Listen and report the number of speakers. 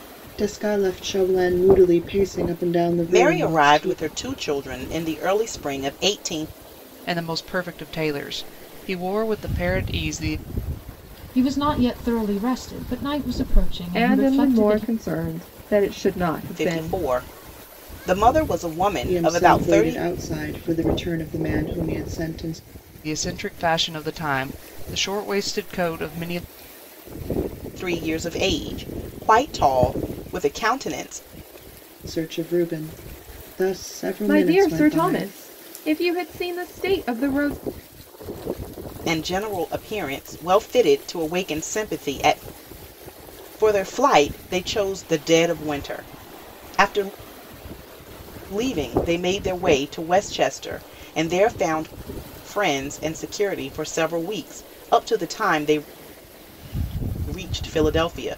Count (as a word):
five